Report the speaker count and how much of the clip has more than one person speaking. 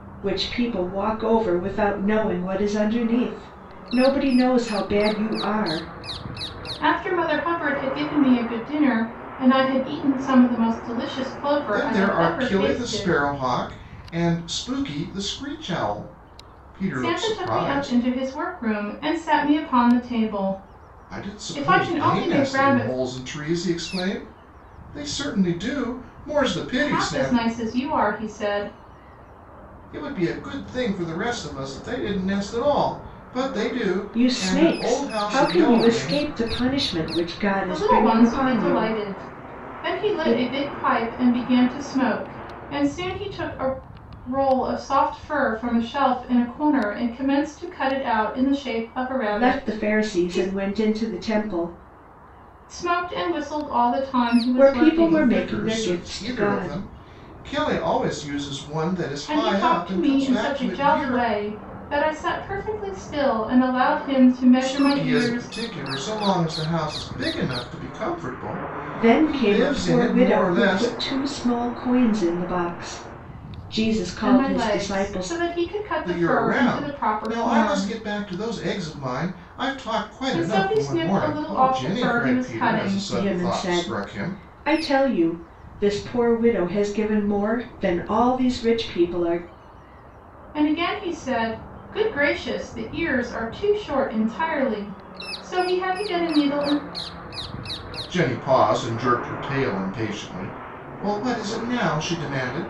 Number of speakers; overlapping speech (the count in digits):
3, about 25%